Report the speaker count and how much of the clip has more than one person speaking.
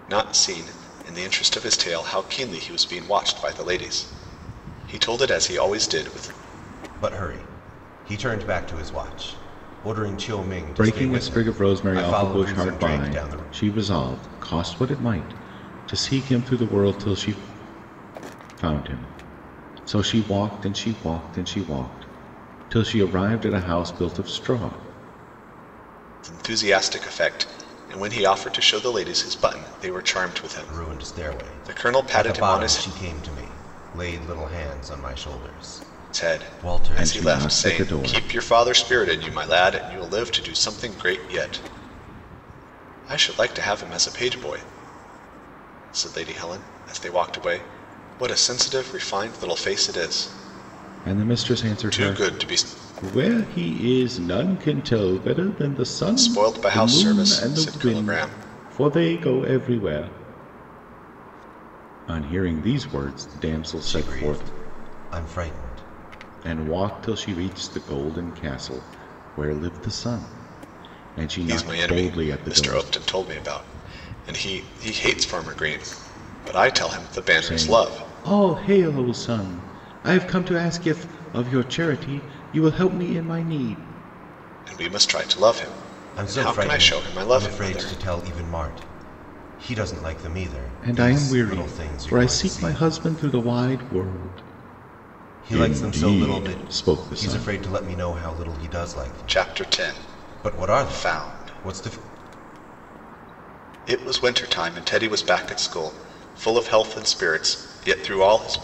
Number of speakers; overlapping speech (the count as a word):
three, about 21%